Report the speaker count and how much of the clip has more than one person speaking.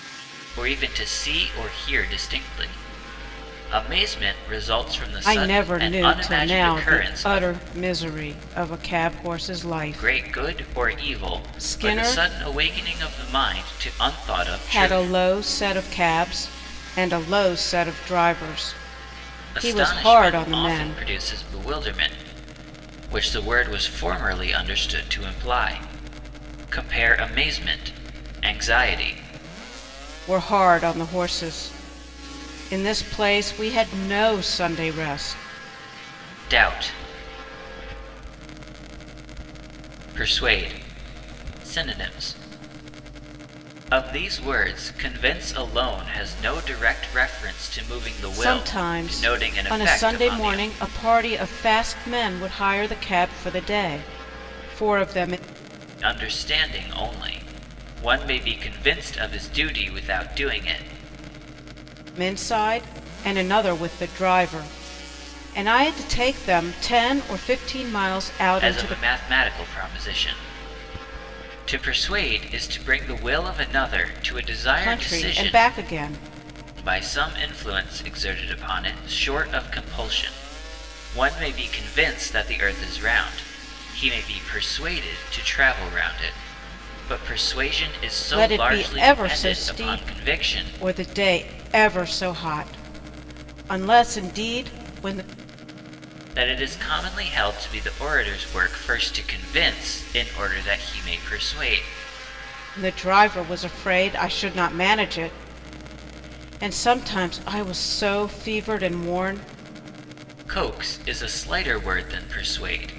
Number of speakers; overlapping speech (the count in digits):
2, about 11%